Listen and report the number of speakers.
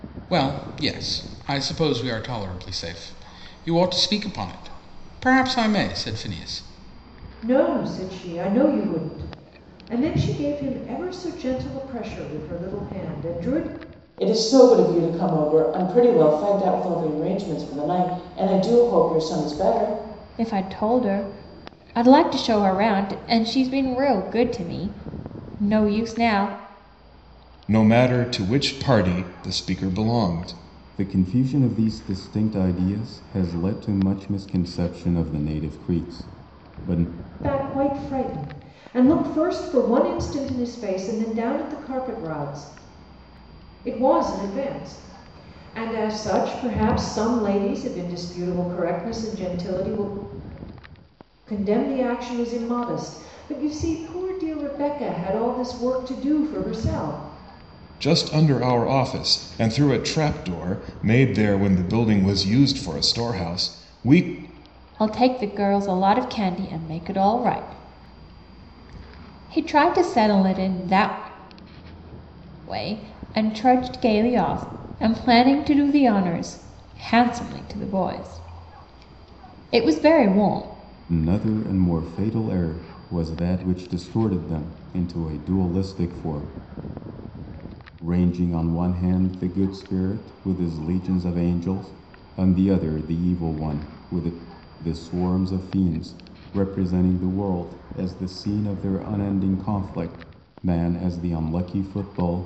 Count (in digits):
6